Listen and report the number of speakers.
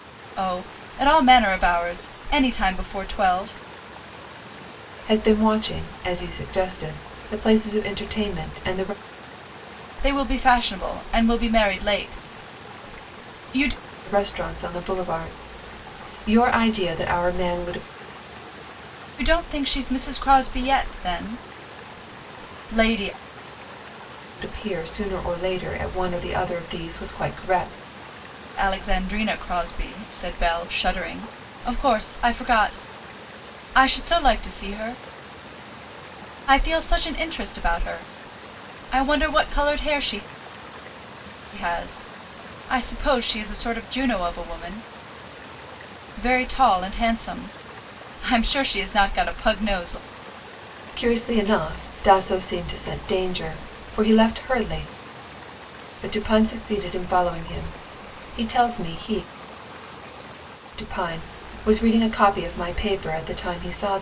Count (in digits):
2